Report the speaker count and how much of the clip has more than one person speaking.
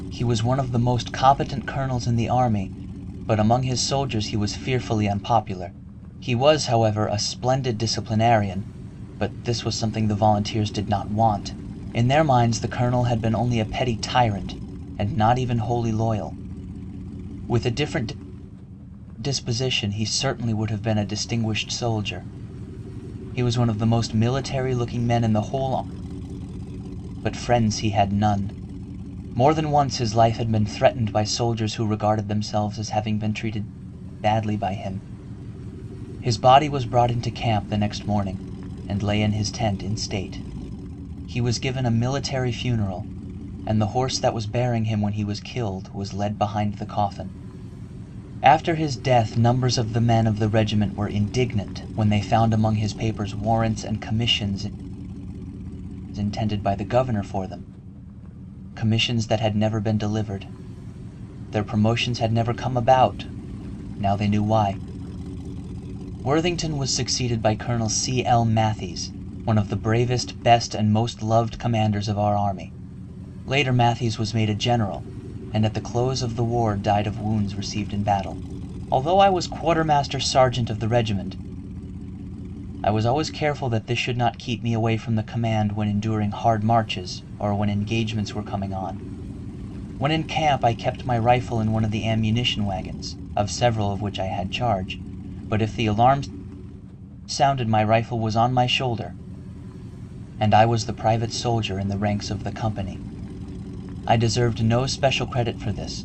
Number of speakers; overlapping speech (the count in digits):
1, no overlap